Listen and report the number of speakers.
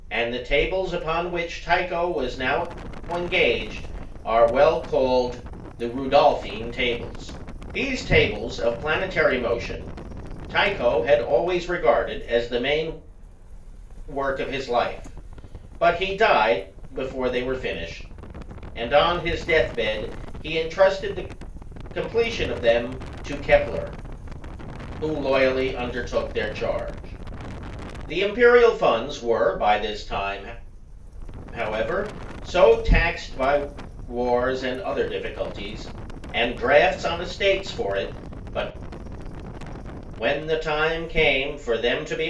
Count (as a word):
one